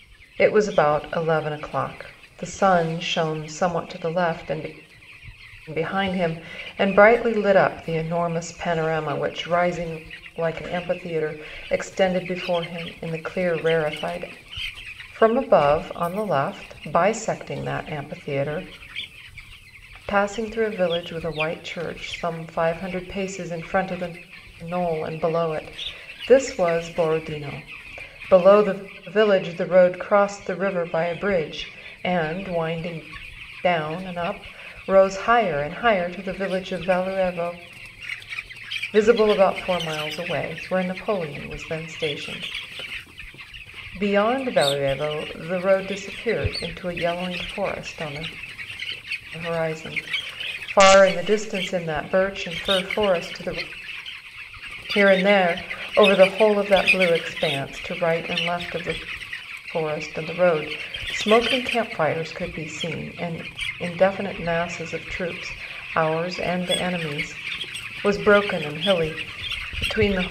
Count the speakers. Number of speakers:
1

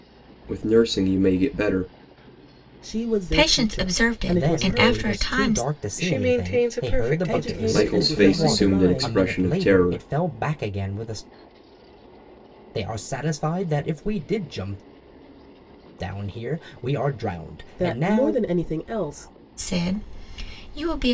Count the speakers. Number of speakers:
5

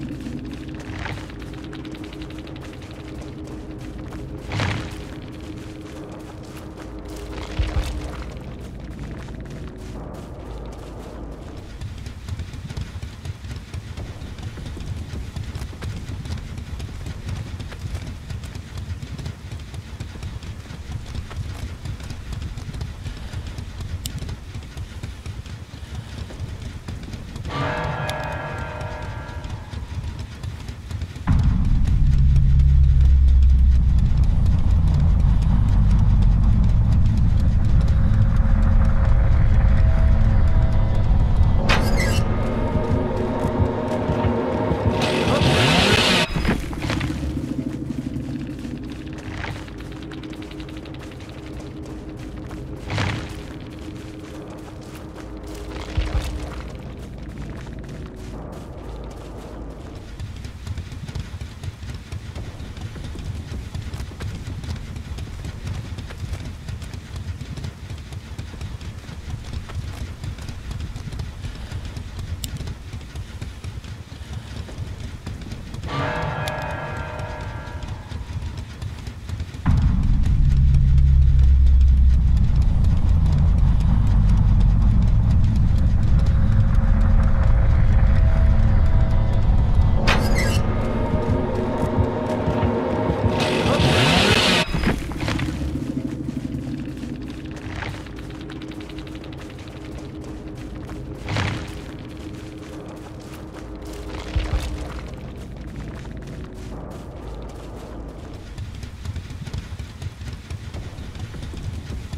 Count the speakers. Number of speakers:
0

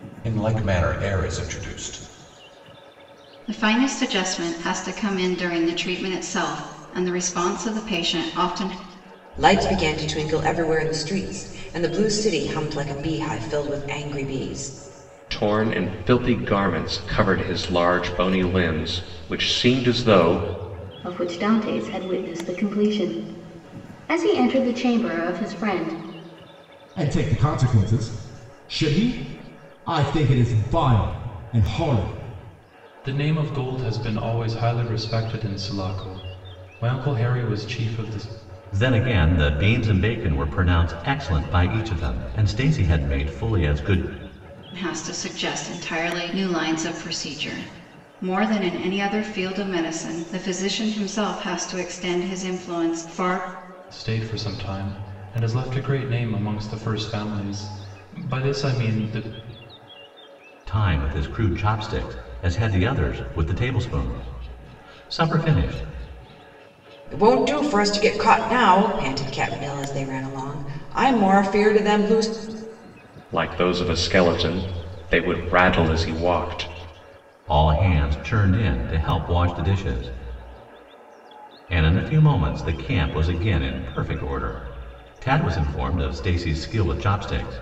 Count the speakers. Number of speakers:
8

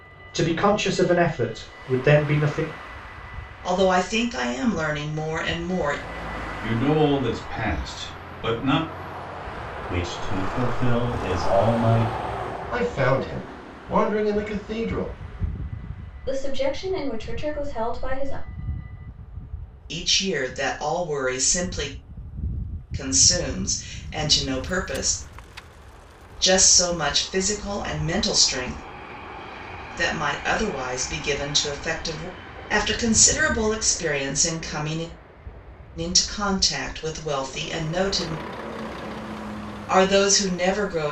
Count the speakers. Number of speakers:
6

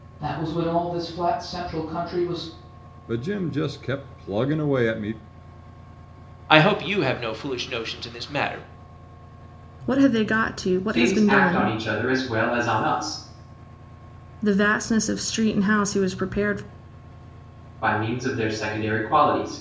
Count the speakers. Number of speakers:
5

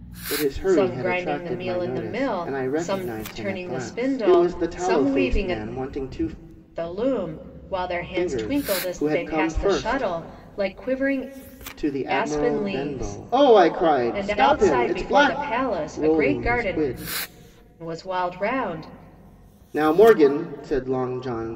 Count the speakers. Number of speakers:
2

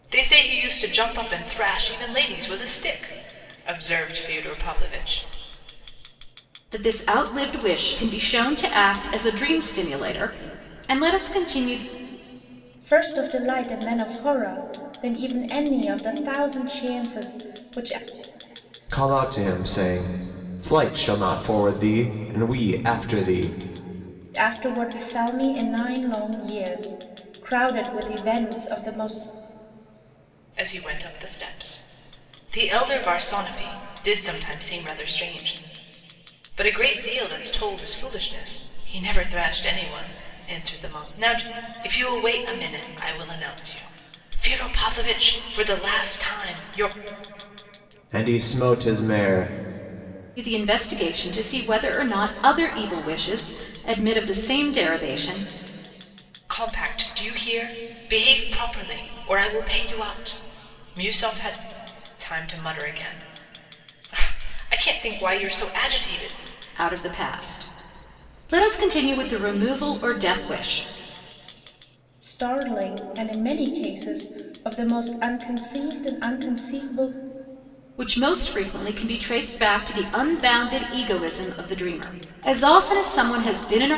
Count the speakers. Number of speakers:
4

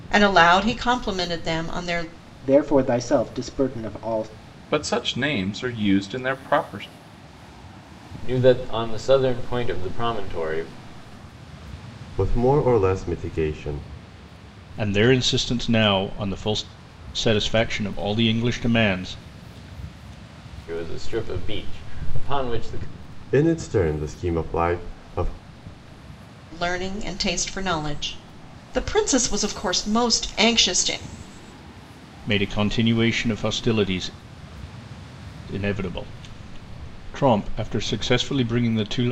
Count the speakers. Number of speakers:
6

